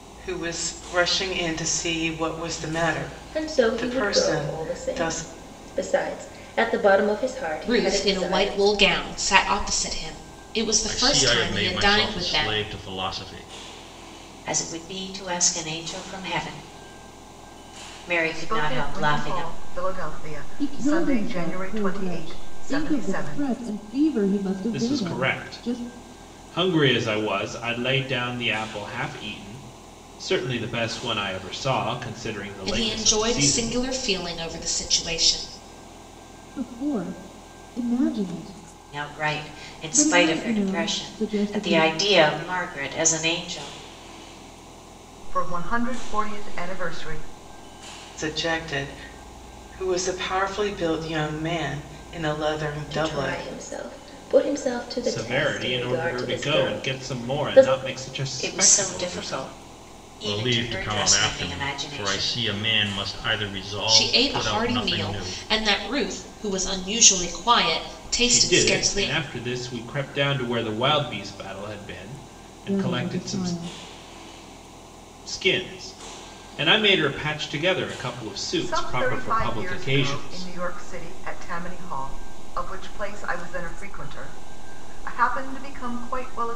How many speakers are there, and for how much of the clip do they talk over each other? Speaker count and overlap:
8, about 30%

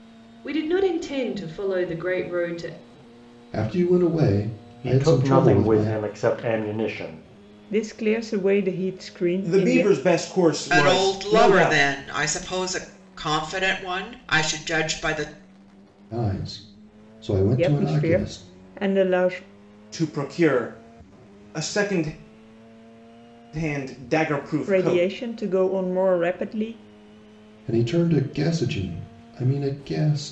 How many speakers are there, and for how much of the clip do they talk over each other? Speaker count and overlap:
6, about 14%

